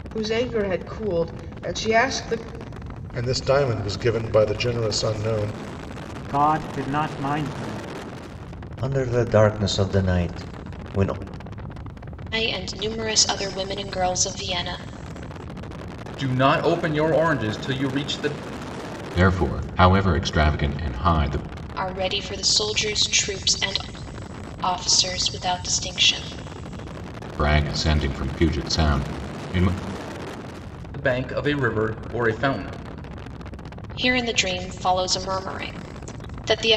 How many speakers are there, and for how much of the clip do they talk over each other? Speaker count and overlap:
7, no overlap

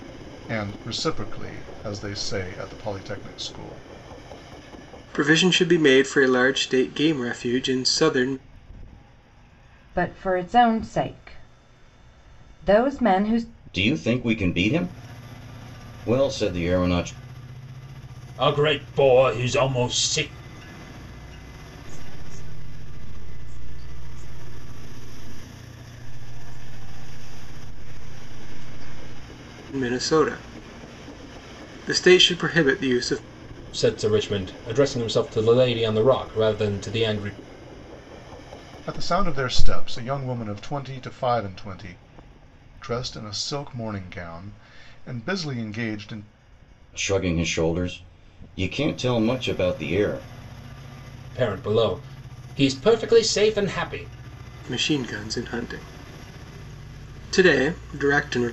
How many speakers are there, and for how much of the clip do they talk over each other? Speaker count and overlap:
6, no overlap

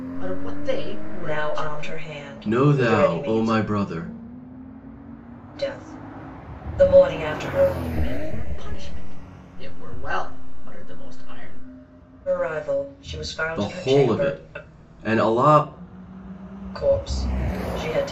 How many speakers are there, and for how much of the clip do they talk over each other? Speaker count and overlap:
3, about 18%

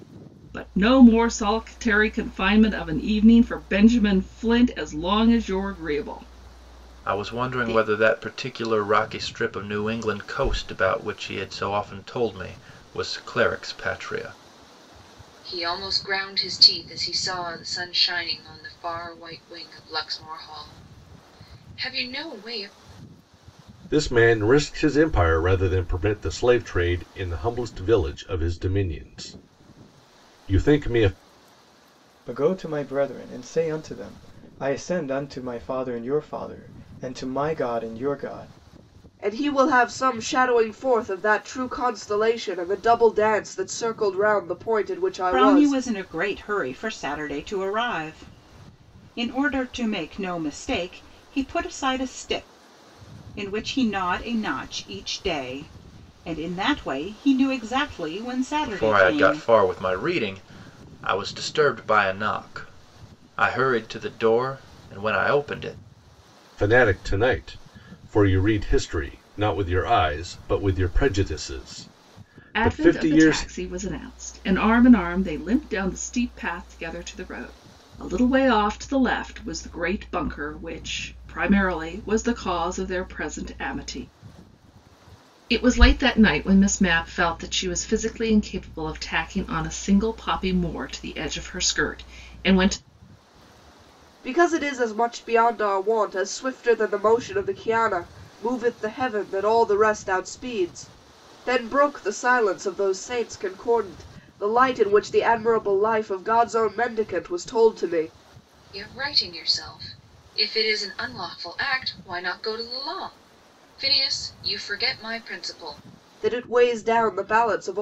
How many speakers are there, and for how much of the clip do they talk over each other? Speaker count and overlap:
7, about 3%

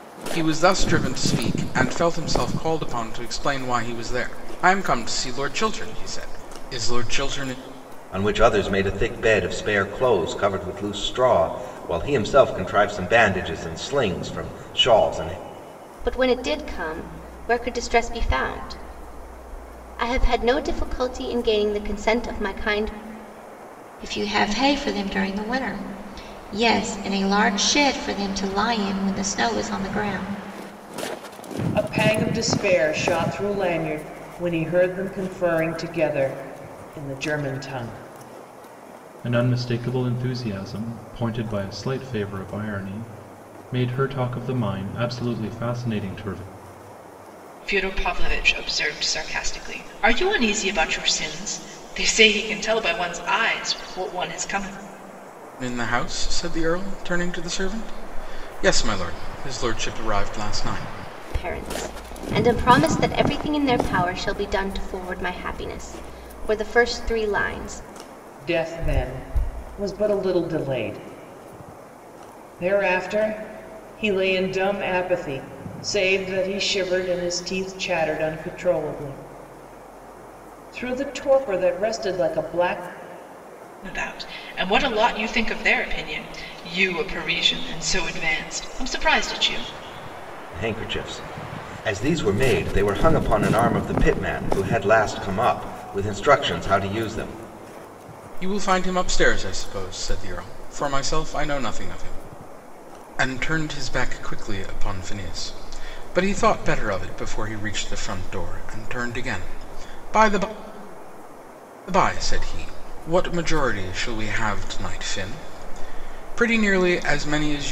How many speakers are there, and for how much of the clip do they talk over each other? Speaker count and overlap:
7, no overlap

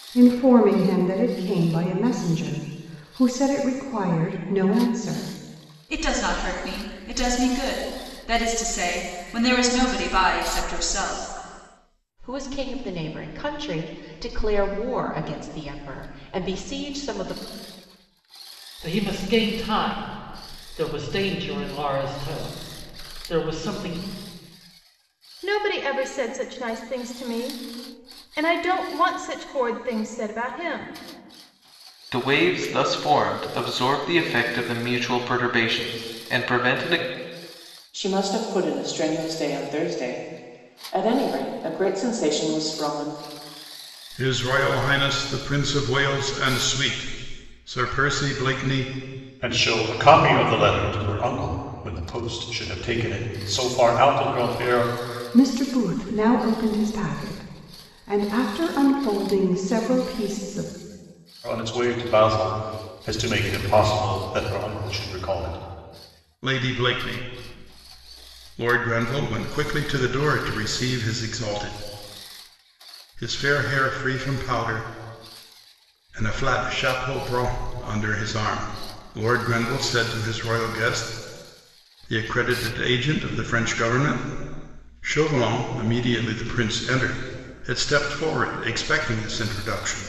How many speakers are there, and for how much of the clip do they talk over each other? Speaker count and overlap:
9, no overlap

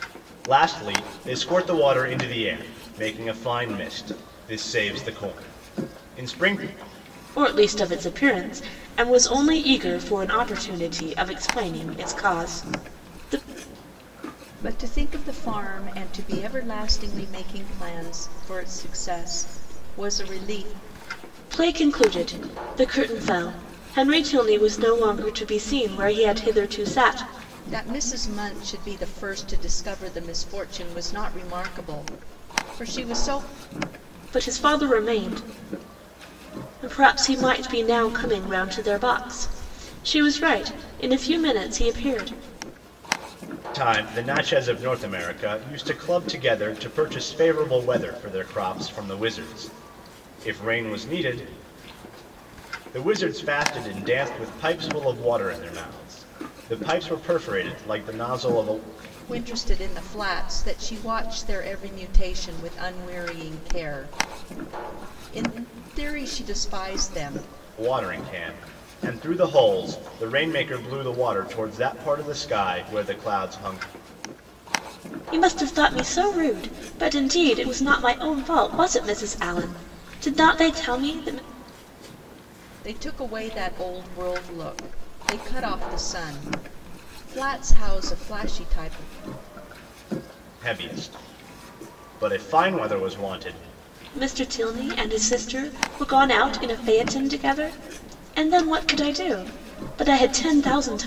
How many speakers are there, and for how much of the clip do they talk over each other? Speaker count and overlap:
3, no overlap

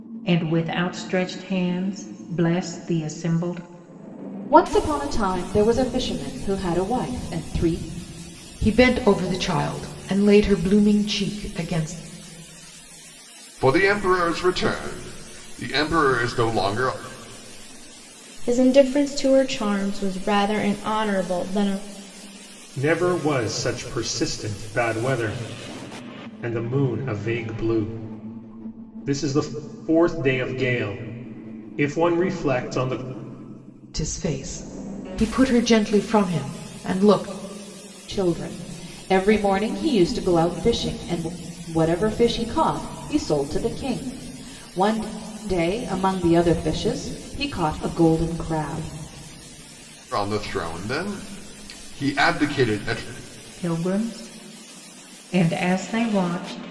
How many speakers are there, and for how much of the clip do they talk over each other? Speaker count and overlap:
6, no overlap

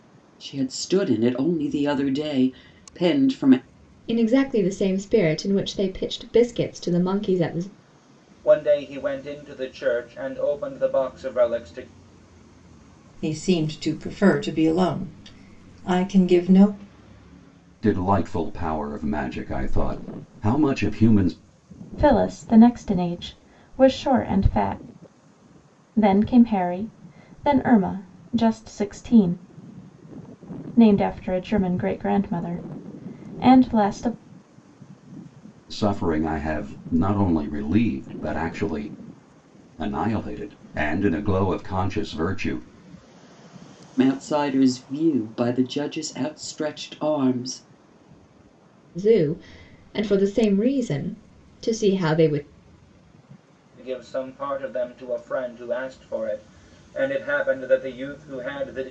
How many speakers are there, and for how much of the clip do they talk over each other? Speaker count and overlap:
6, no overlap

